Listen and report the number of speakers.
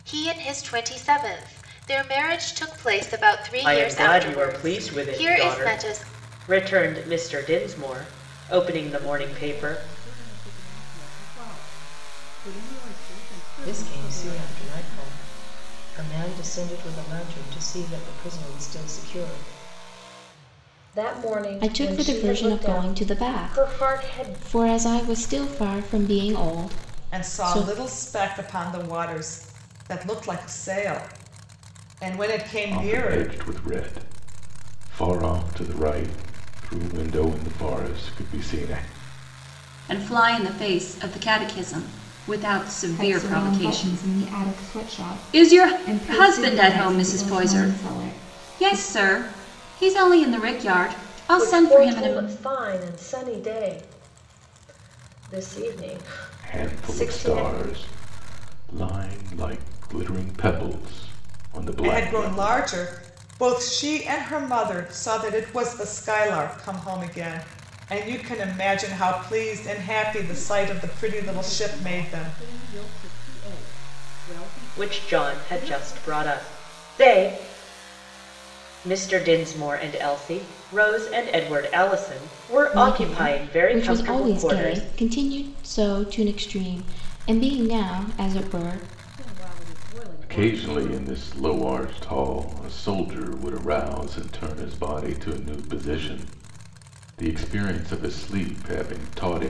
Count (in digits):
10